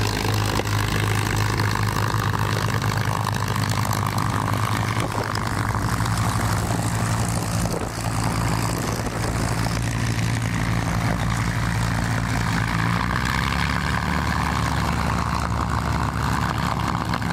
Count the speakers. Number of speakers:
0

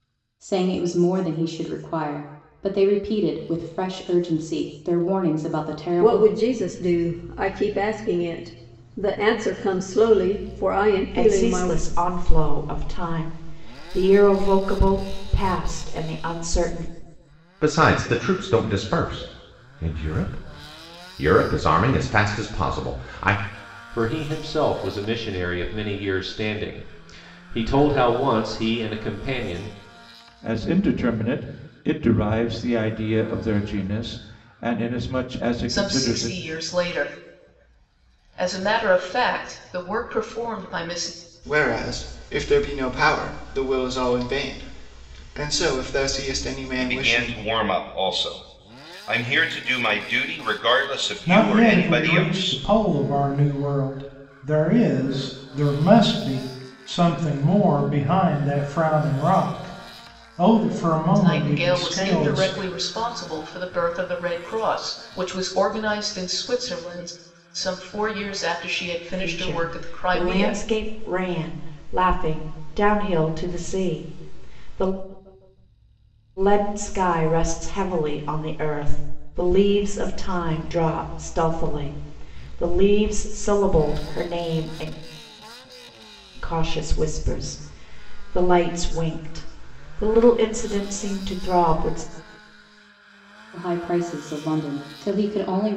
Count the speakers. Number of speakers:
10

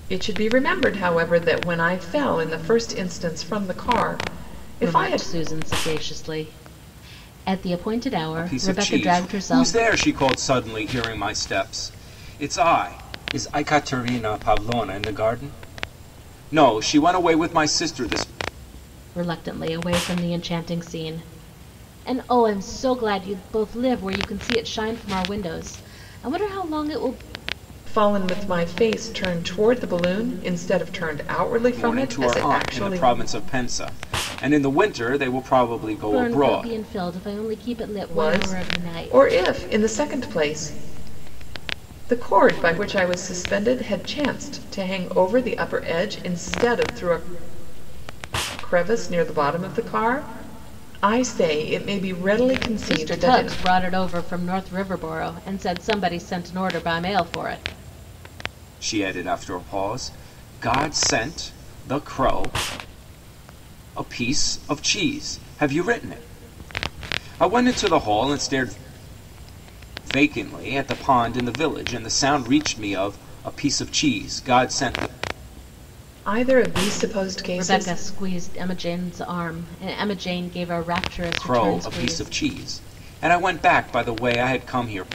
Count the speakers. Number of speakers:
3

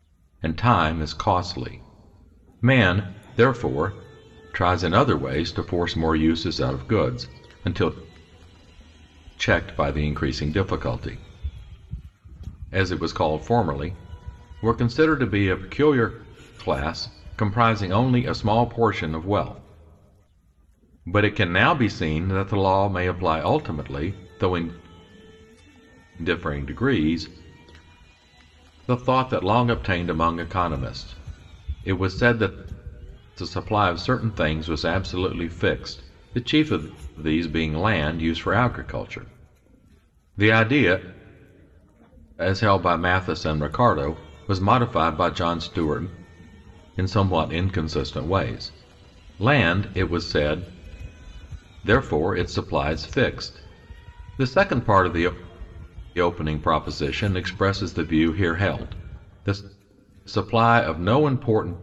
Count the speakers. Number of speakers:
1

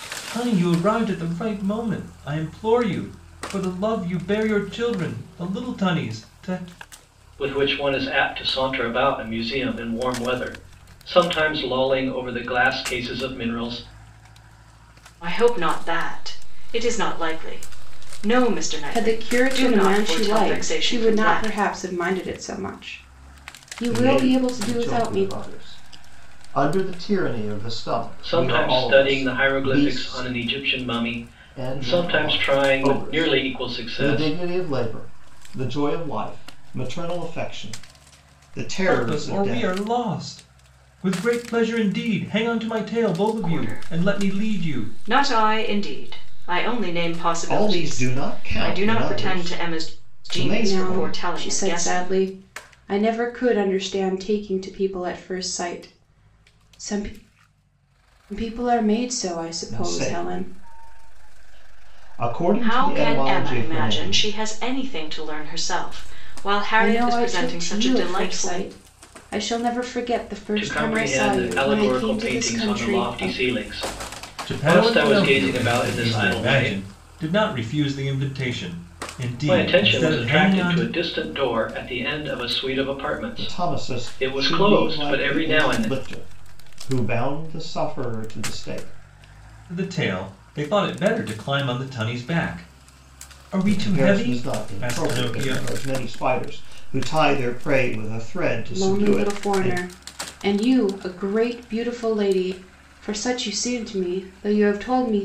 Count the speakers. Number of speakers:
5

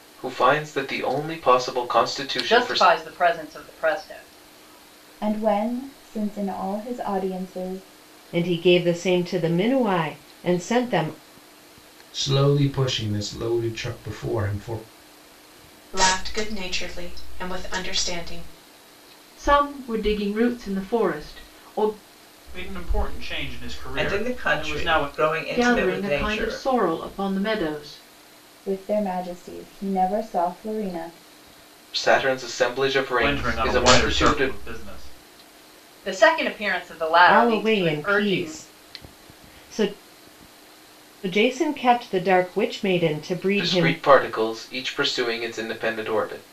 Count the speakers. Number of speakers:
9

